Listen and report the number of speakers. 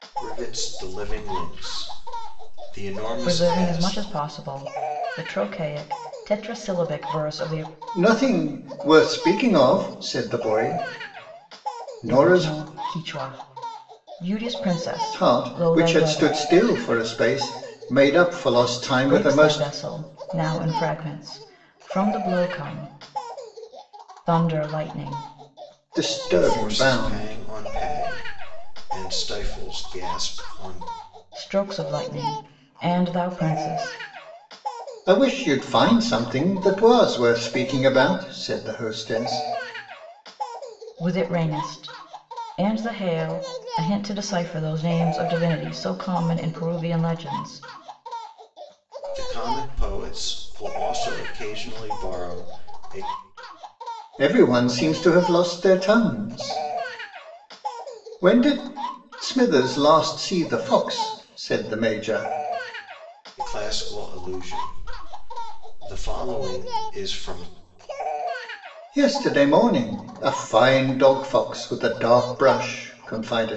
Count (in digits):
3